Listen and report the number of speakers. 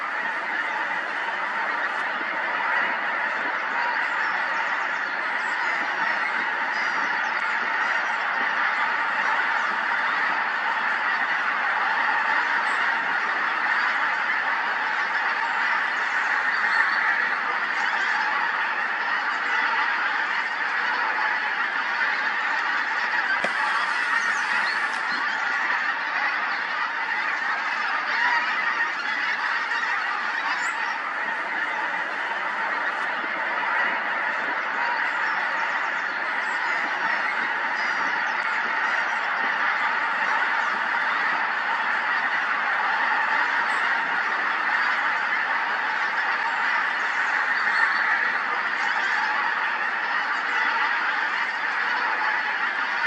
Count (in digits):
0